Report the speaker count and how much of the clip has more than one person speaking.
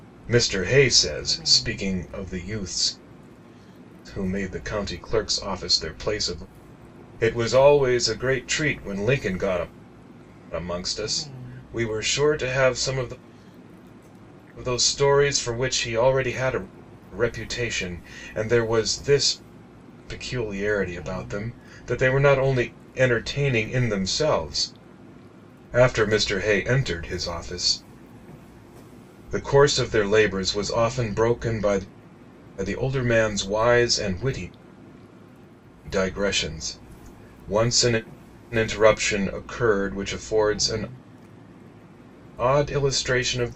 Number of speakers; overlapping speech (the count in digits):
1, no overlap